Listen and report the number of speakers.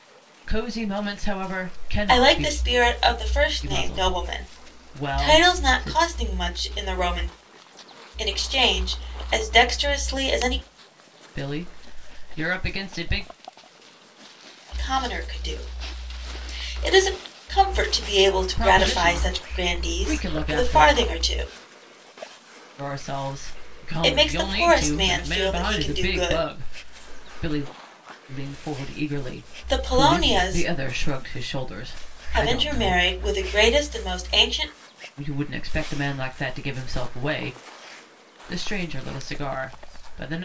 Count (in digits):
2